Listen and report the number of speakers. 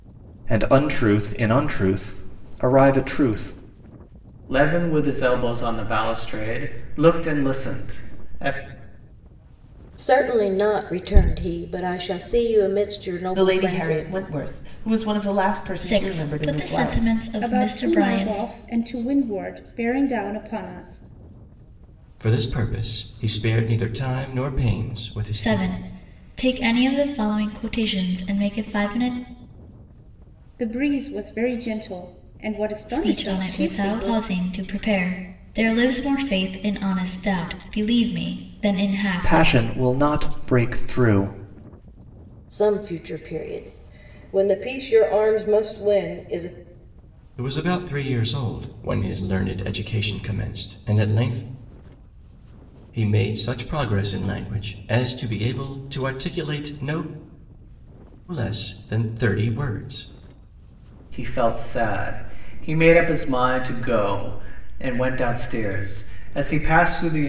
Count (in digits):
7